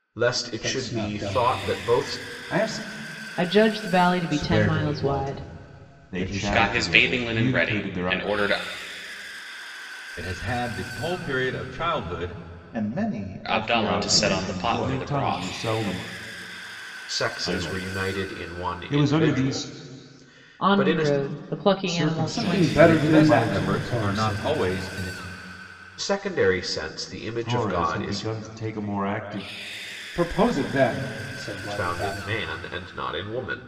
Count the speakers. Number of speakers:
8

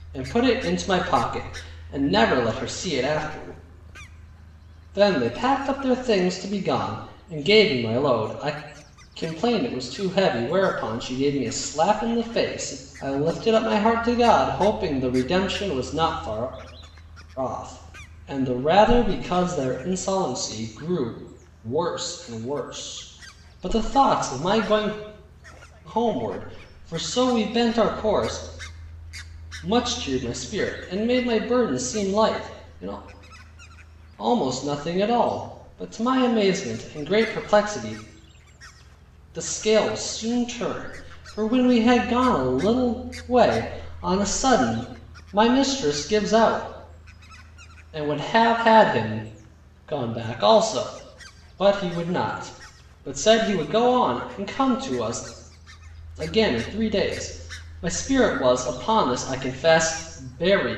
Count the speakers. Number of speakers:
1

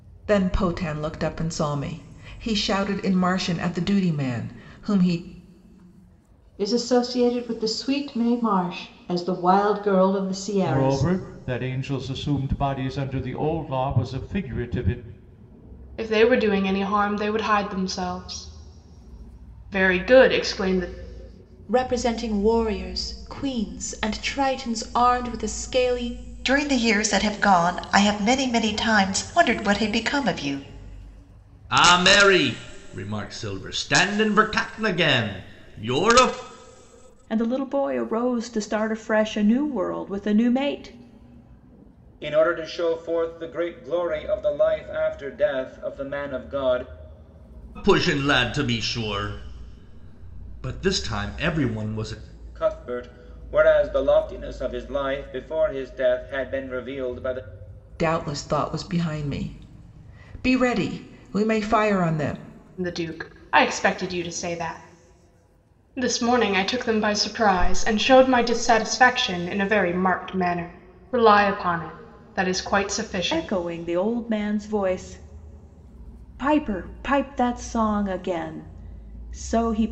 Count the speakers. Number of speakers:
9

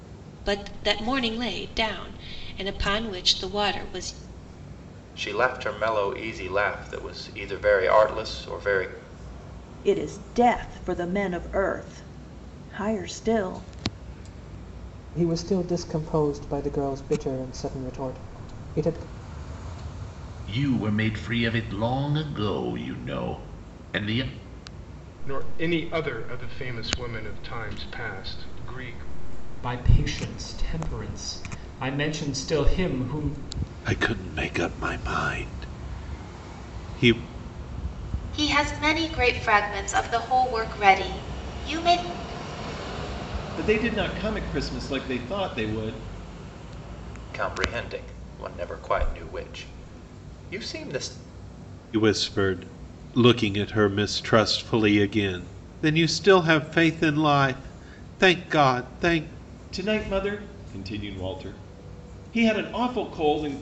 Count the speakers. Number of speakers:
10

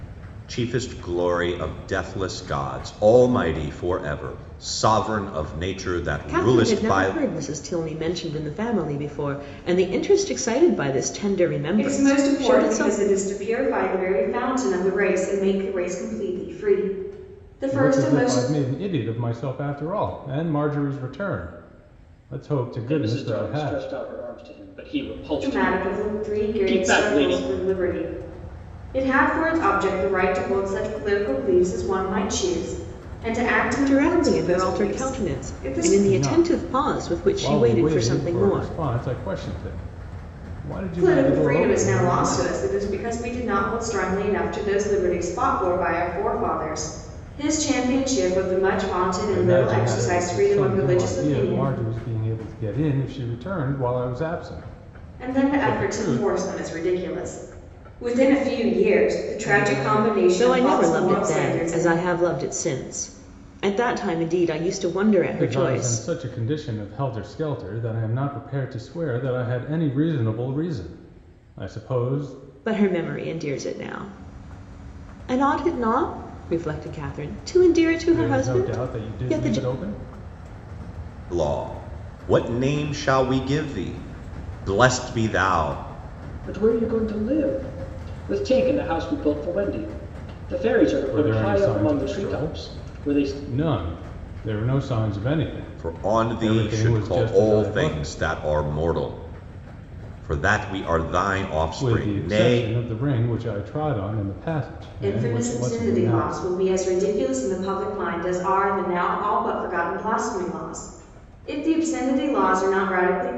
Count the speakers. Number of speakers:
5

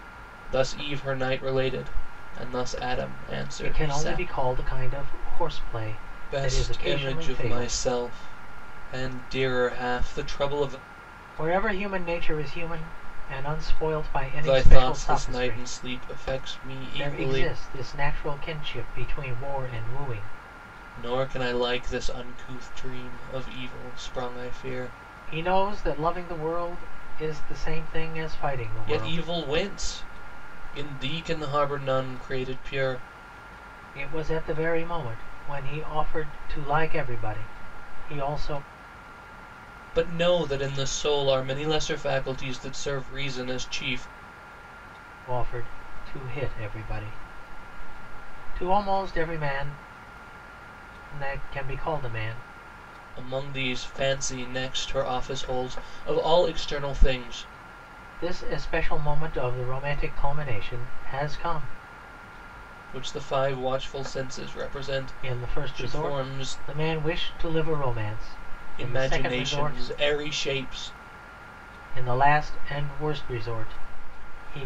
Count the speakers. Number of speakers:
2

